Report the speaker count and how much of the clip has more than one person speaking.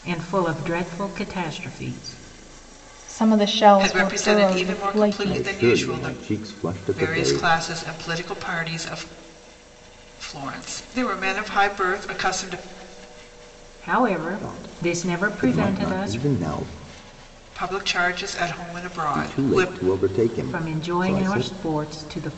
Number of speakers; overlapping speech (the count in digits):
4, about 30%